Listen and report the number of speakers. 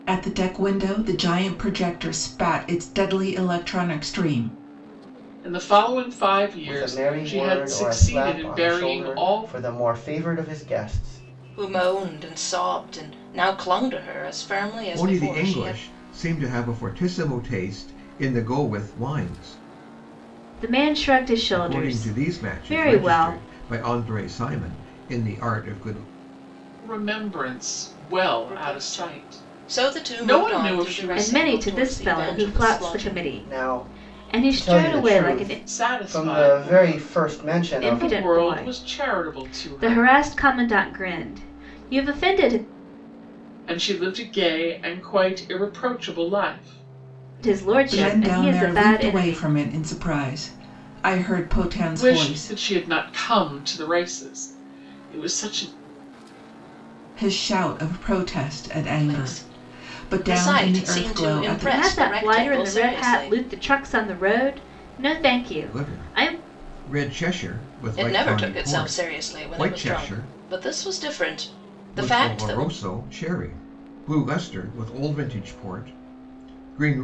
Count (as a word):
six